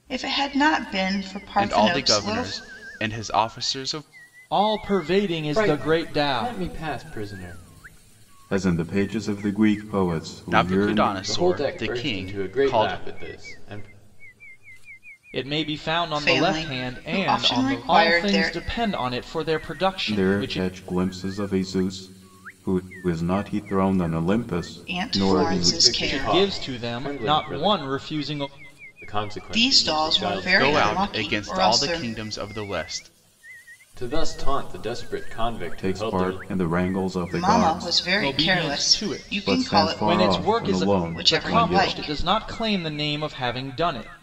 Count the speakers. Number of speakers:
5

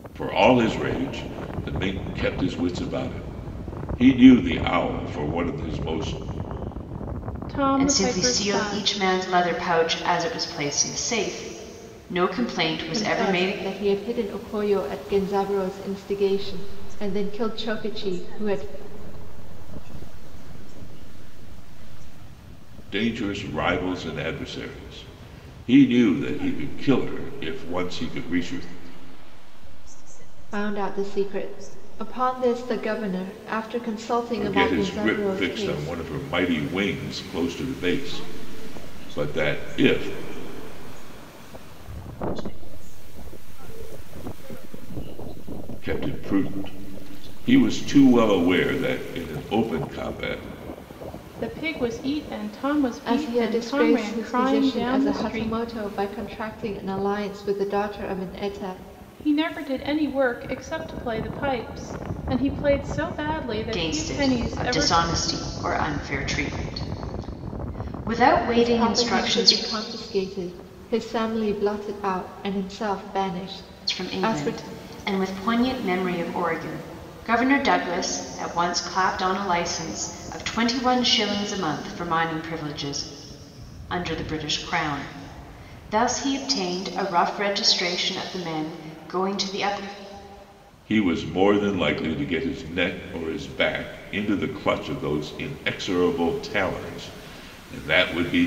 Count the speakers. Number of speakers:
5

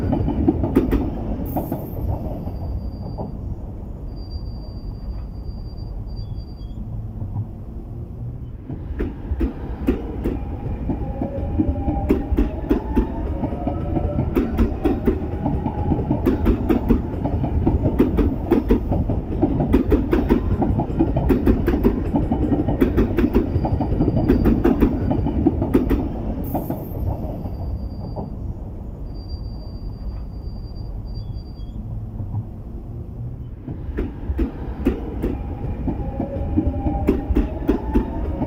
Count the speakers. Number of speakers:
0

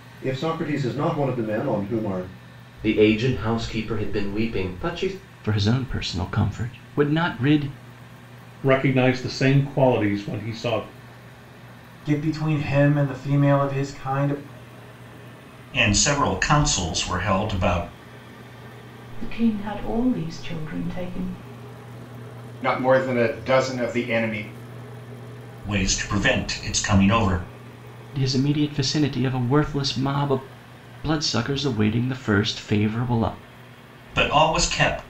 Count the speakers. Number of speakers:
8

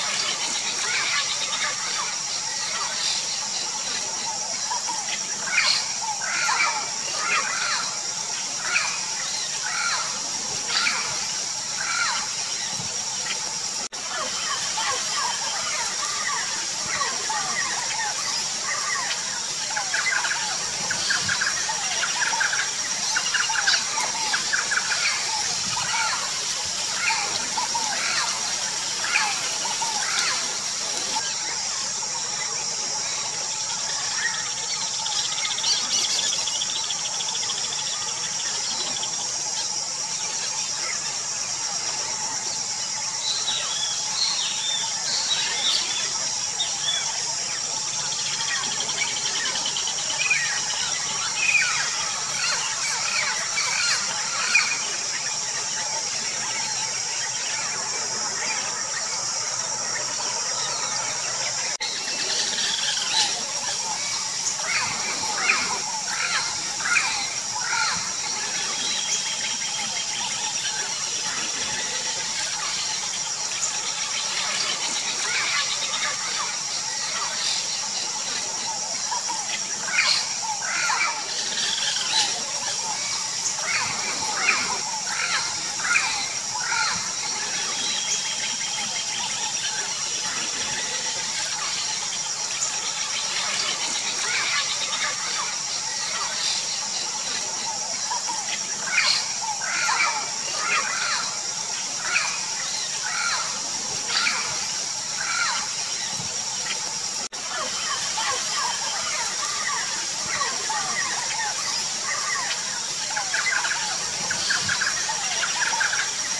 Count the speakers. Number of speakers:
0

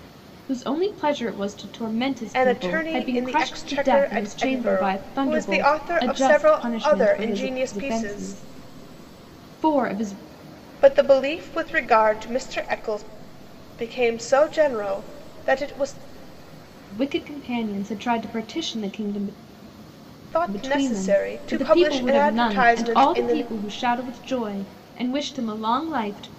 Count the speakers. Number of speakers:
2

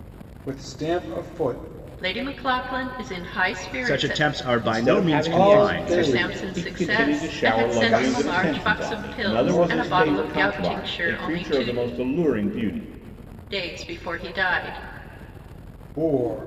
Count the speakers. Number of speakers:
4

